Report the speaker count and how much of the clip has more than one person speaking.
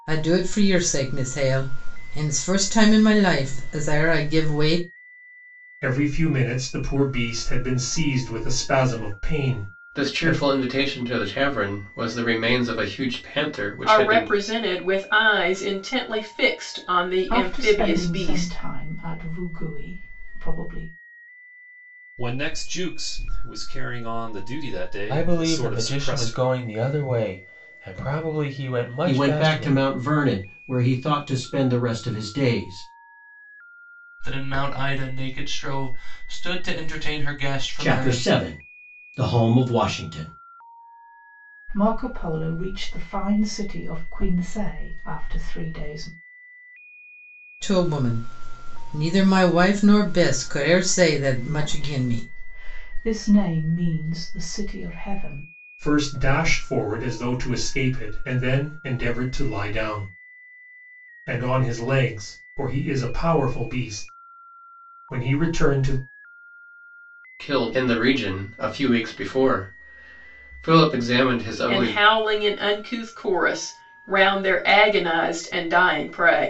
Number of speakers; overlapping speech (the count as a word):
nine, about 8%